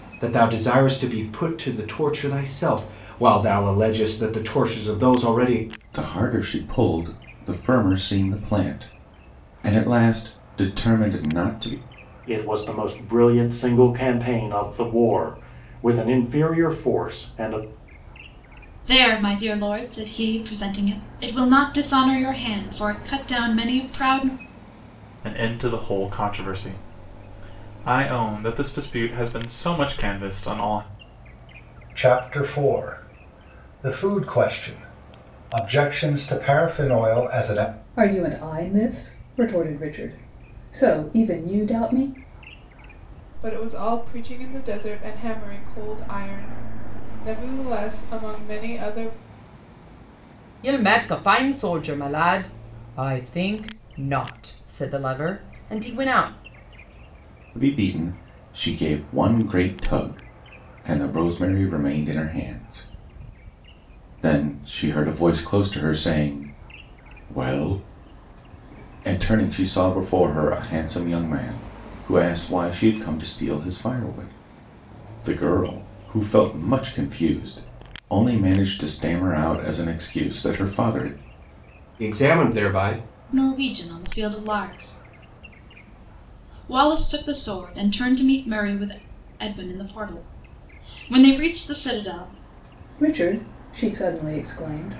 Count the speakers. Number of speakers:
9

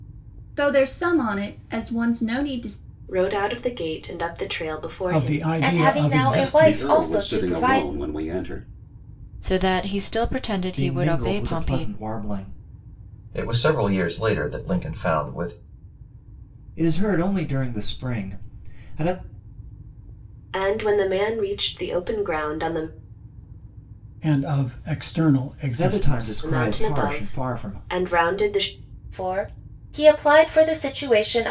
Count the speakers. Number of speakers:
8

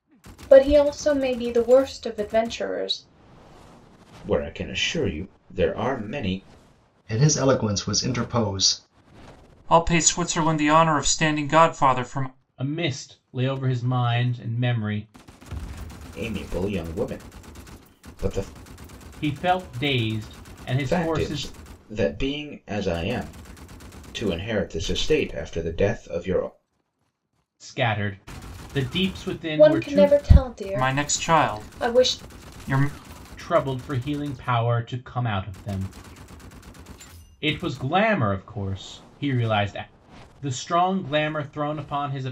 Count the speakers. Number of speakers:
5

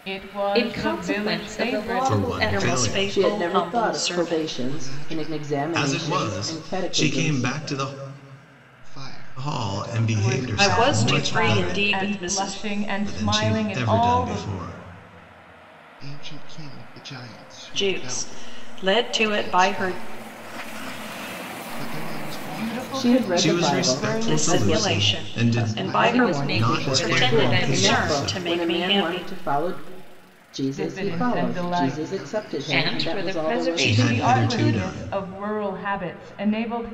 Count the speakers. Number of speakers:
6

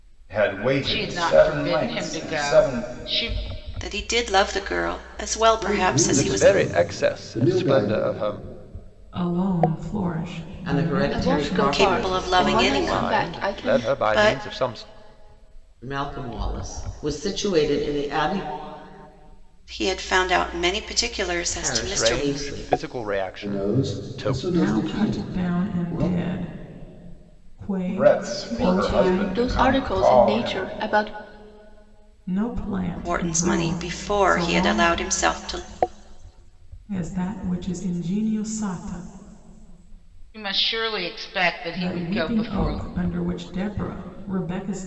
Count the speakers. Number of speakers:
8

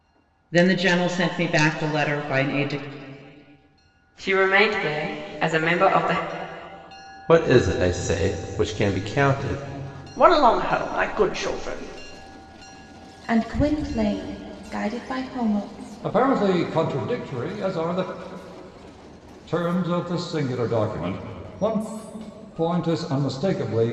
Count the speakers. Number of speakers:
6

